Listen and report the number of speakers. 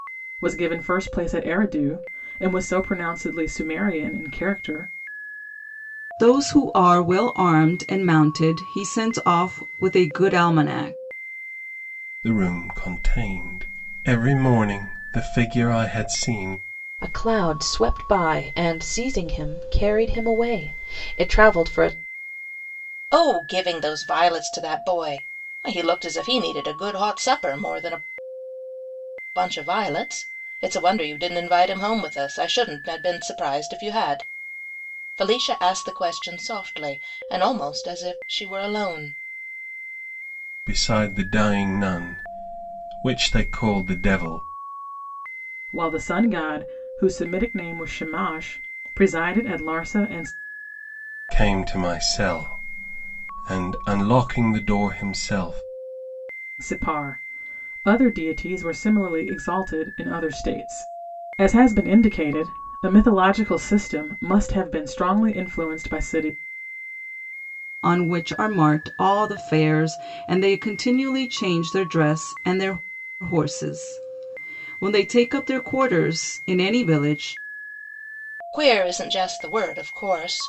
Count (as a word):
five